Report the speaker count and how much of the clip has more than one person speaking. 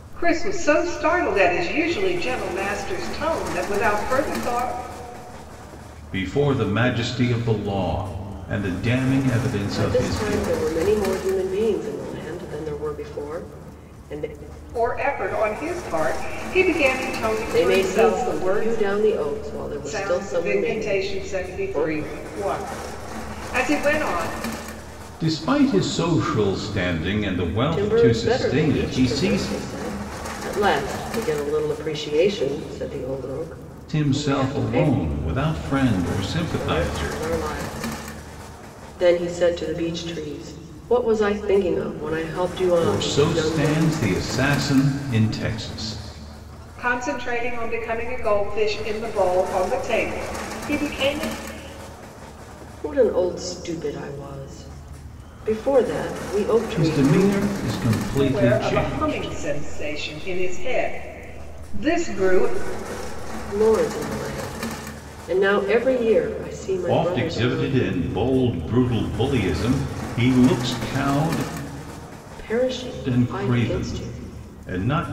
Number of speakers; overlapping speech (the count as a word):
three, about 18%